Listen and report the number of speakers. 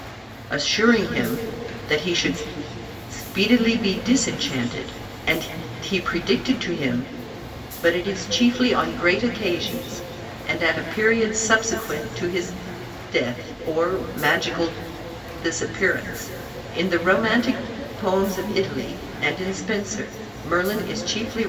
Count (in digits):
1